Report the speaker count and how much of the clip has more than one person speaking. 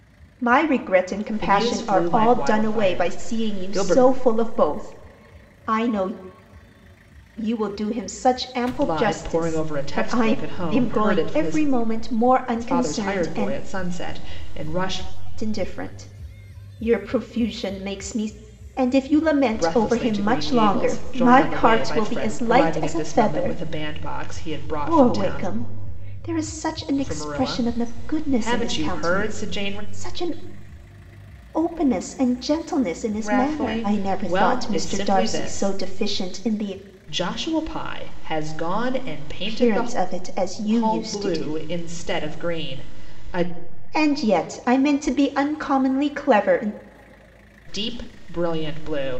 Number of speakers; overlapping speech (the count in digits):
2, about 37%